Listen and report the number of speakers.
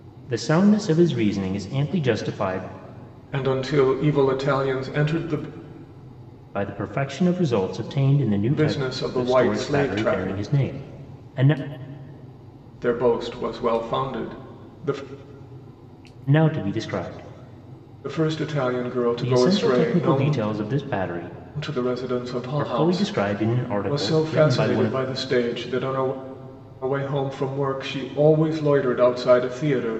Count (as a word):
two